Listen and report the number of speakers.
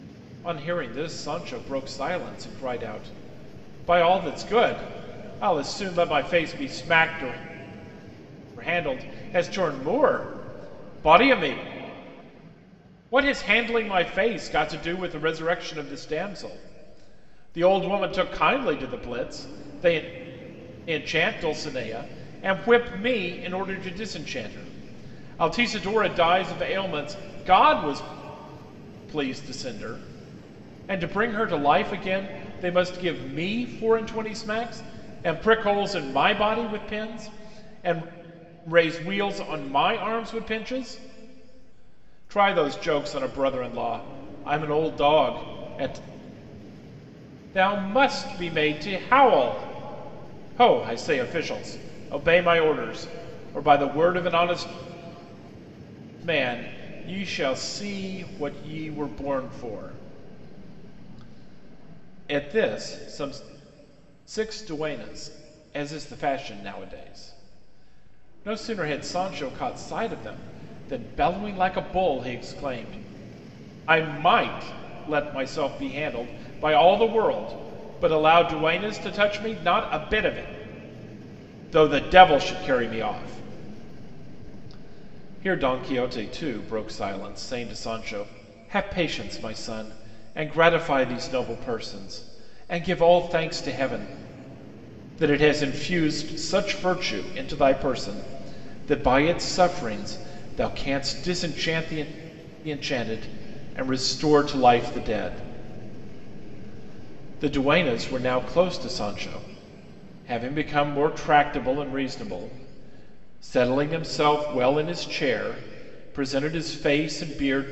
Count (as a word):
one